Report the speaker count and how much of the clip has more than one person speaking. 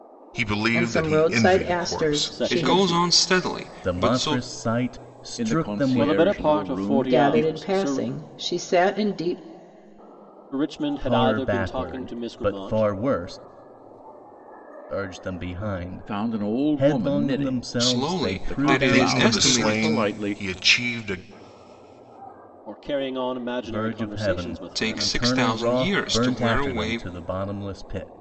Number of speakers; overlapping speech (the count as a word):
six, about 54%